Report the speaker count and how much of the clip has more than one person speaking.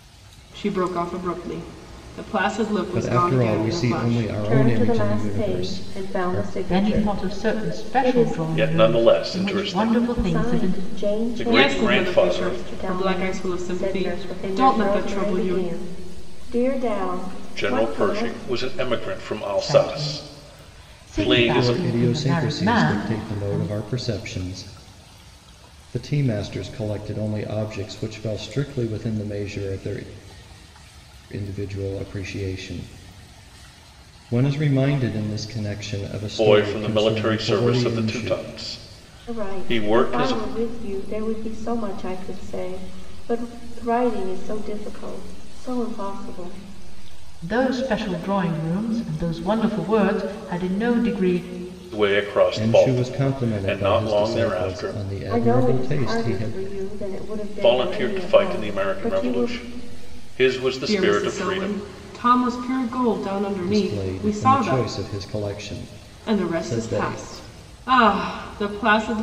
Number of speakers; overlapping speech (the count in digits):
5, about 43%